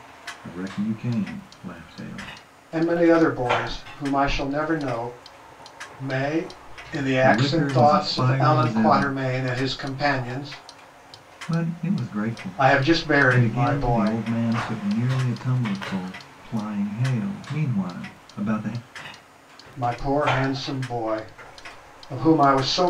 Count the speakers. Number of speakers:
two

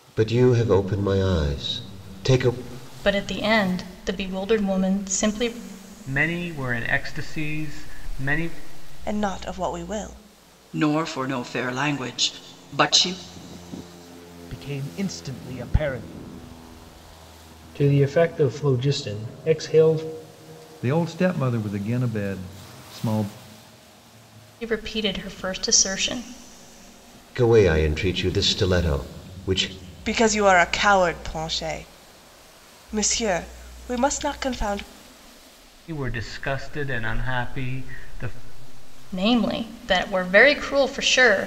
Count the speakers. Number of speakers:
eight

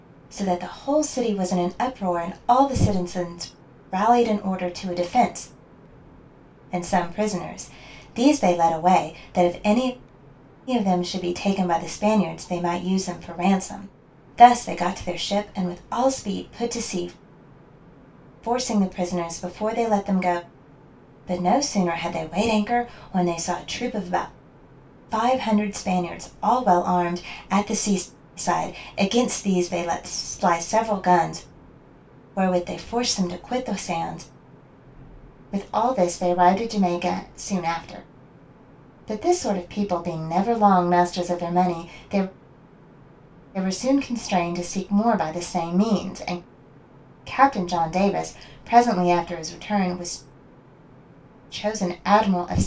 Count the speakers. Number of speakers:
one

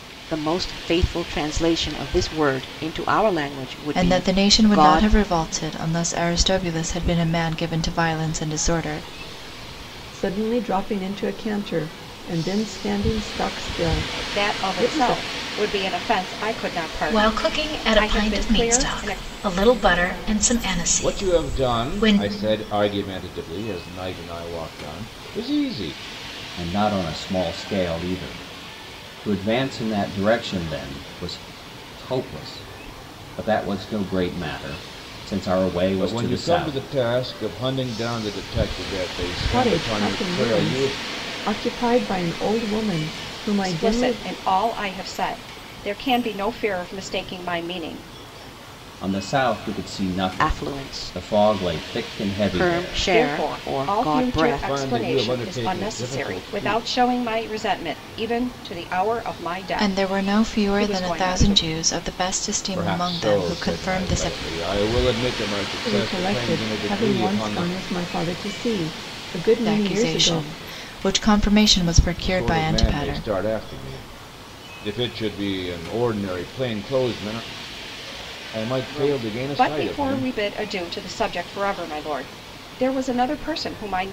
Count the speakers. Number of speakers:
seven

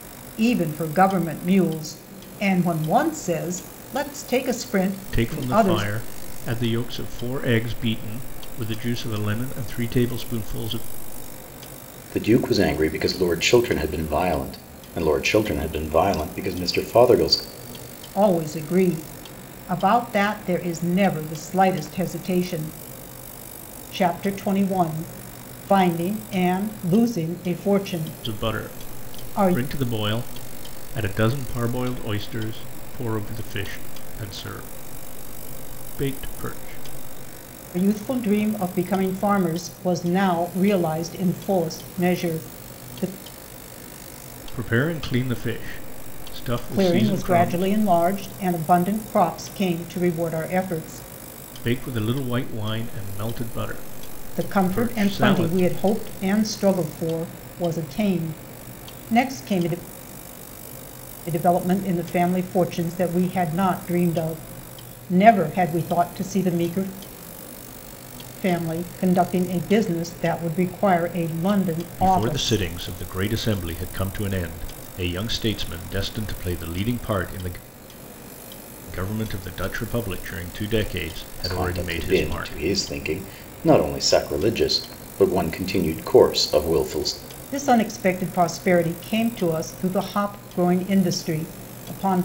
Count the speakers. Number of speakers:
three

